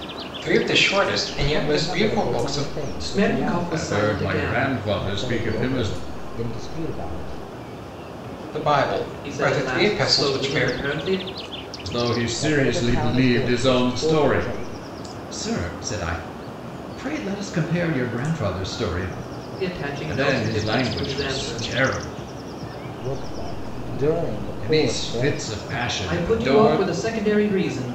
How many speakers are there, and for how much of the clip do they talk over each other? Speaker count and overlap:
four, about 41%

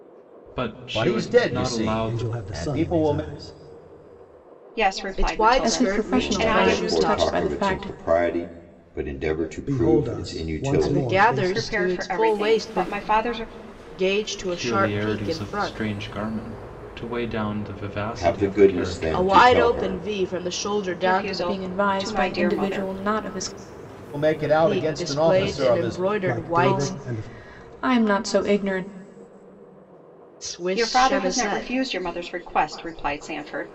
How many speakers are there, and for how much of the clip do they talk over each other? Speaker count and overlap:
seven, about 53%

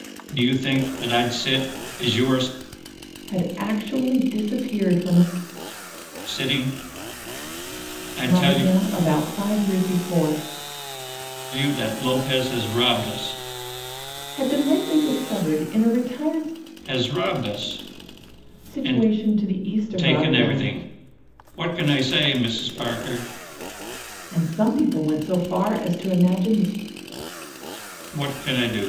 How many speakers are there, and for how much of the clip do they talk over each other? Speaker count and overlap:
two, about 5%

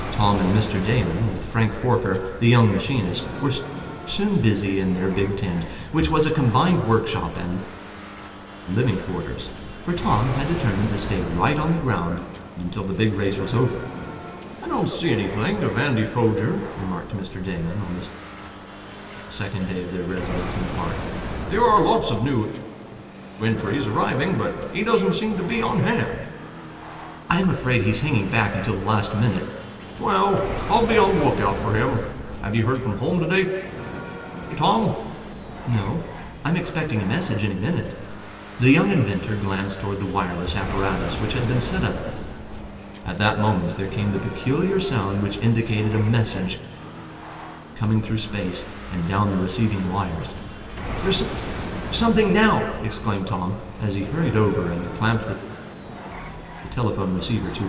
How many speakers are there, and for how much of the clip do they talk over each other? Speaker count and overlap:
one, no overlap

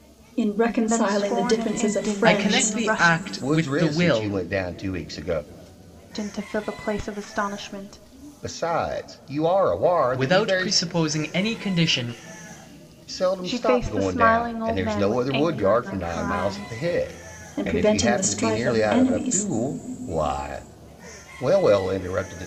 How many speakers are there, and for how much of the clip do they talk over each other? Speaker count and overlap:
four, about 42%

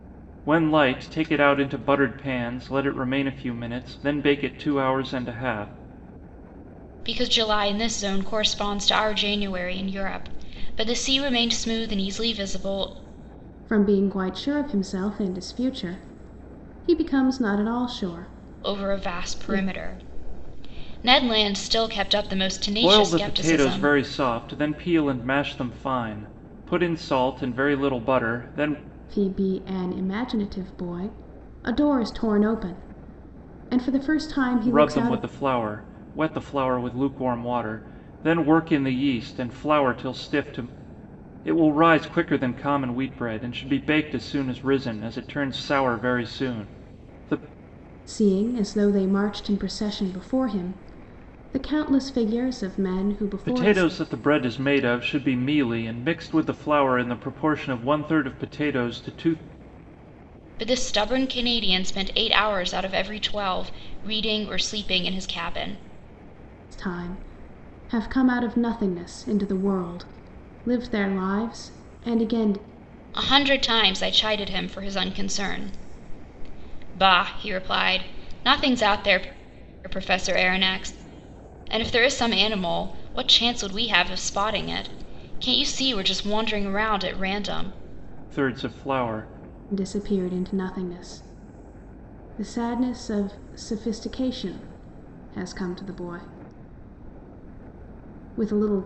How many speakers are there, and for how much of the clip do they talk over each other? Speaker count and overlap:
three, about 3%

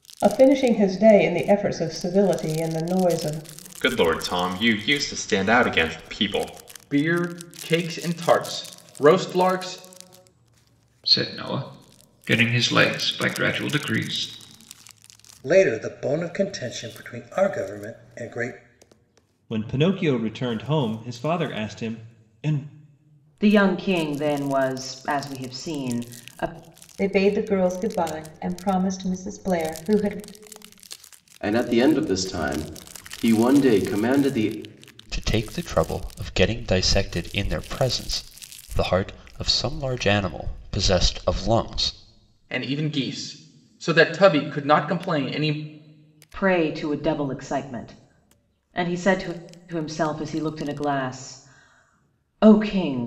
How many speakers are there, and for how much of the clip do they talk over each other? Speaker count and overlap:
ten, no overlap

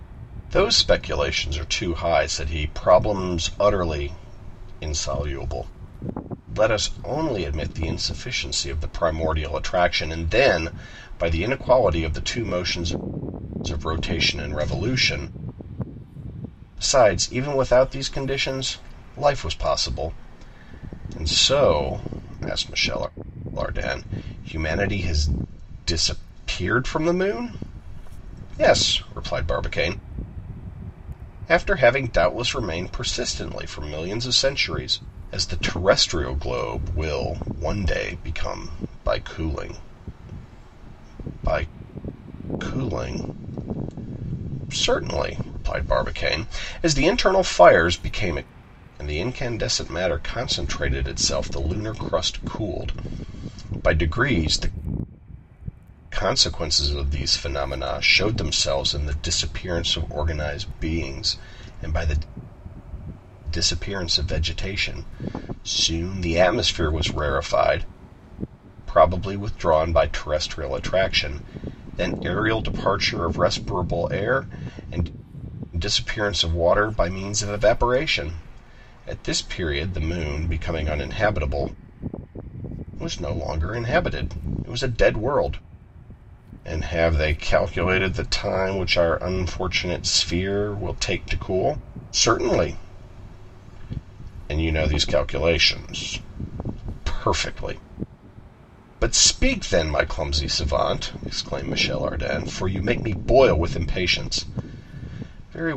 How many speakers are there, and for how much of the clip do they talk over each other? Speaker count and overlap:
one, no overlap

